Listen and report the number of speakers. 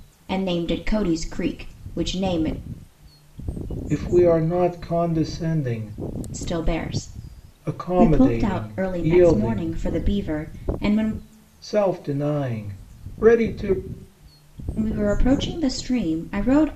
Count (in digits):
2